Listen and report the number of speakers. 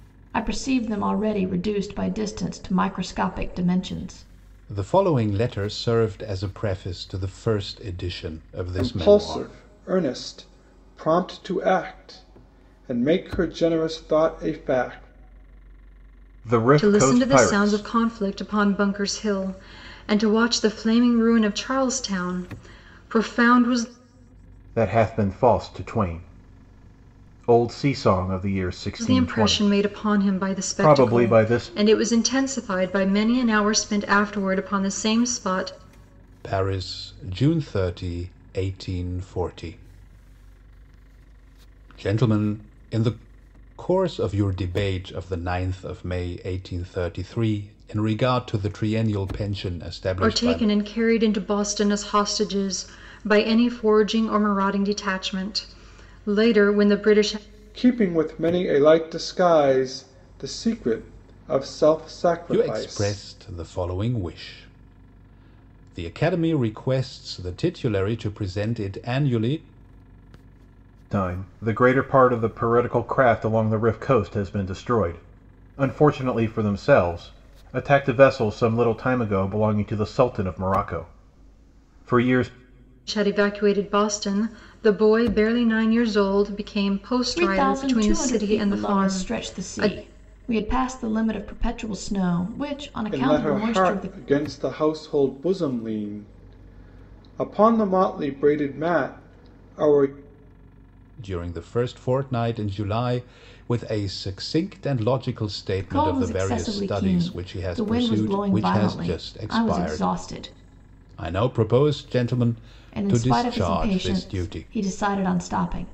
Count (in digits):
5